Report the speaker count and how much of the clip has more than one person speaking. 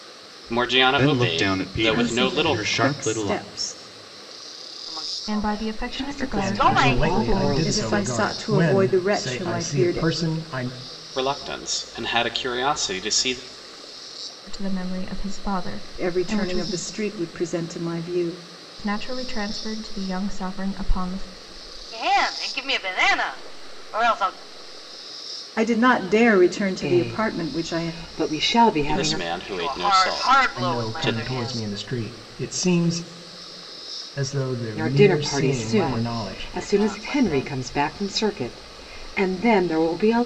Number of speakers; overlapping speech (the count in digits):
7, about 37%